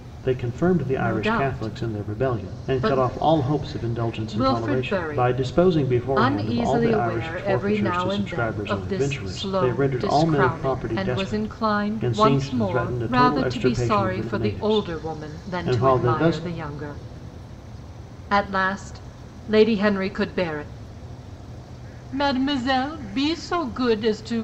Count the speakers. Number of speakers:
2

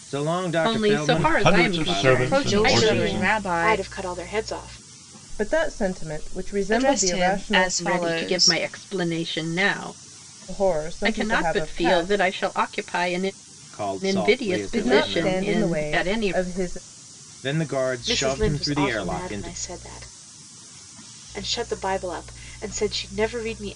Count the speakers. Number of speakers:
6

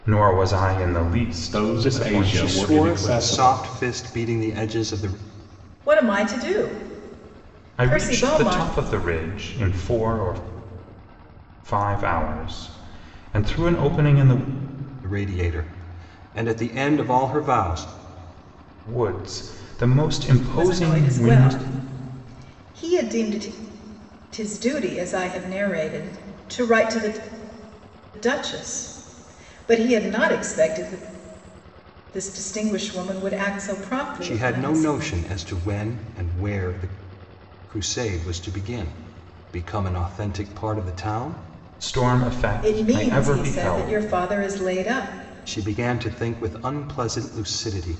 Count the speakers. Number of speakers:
4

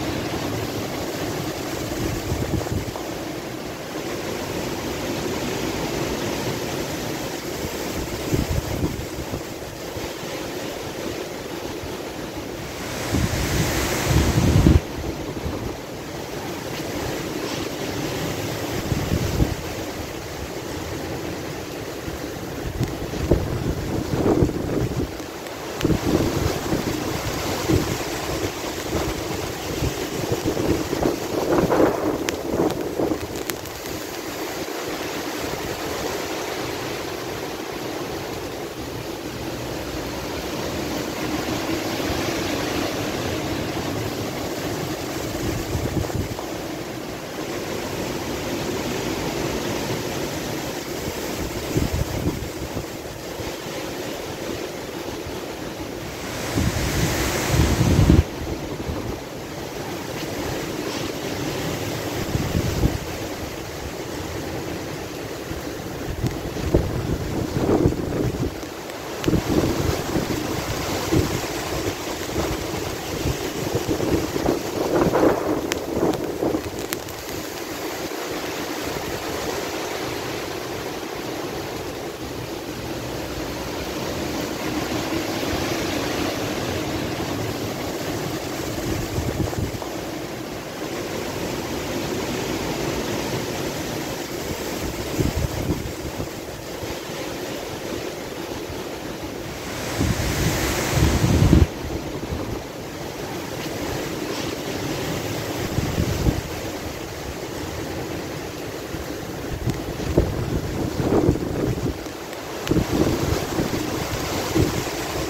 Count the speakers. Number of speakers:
0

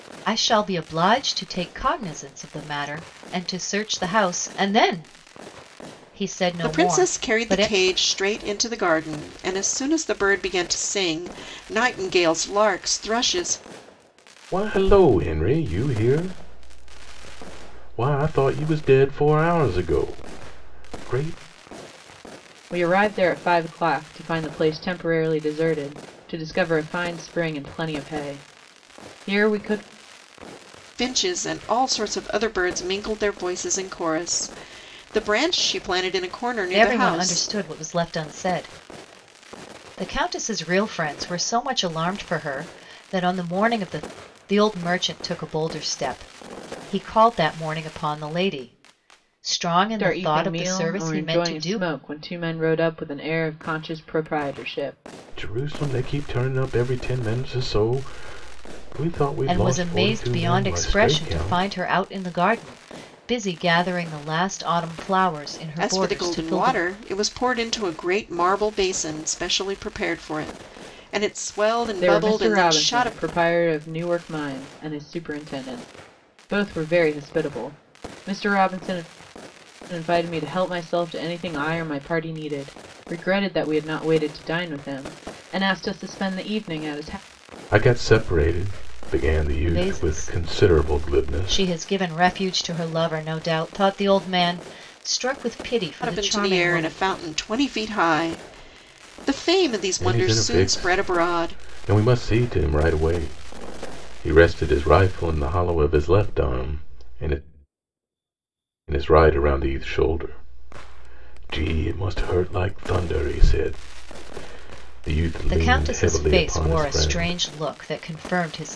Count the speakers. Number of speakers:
4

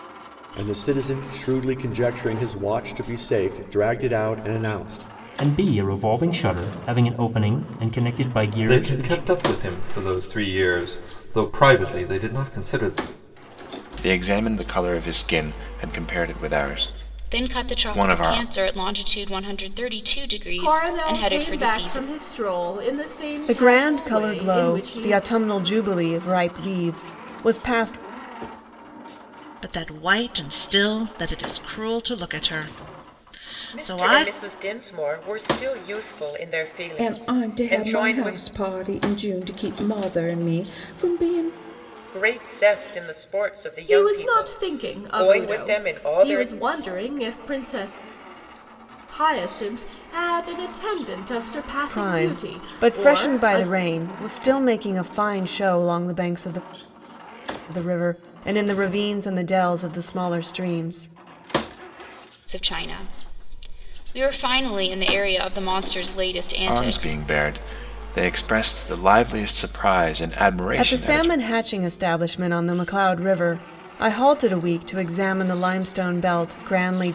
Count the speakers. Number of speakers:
10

